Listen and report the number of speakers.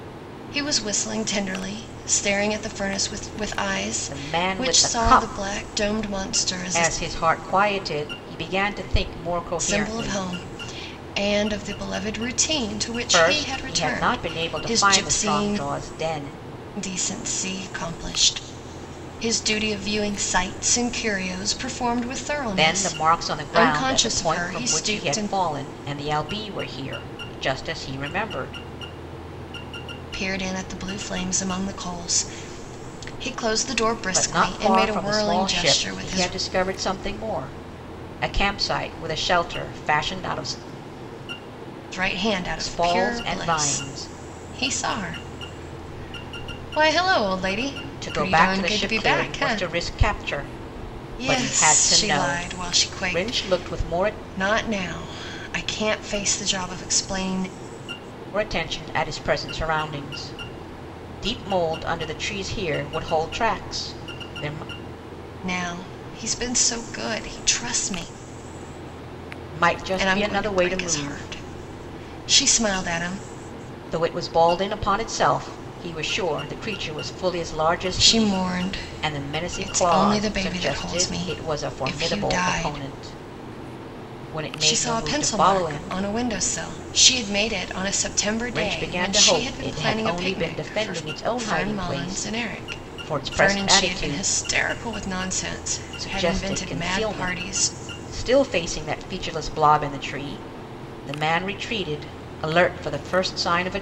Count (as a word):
two